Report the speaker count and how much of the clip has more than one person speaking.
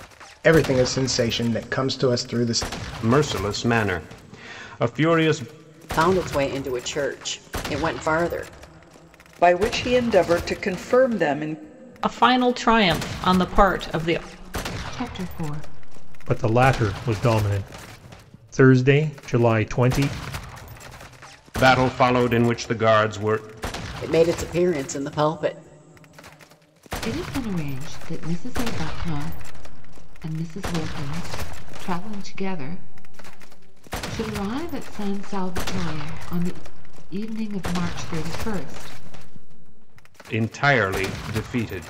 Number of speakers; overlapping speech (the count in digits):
7, no overlap